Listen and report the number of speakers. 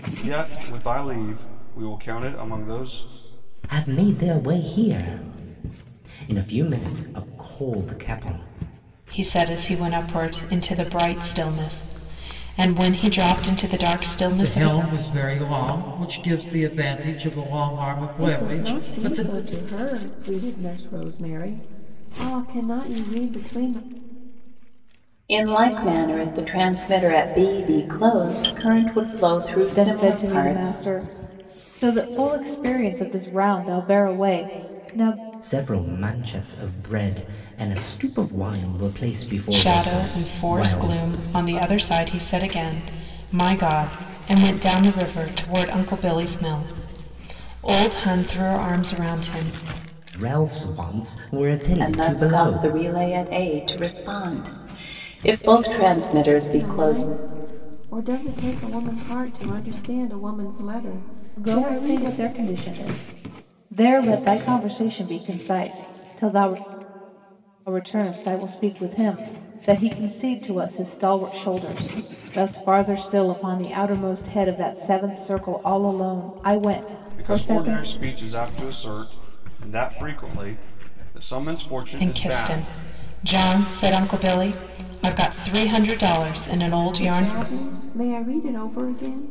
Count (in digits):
7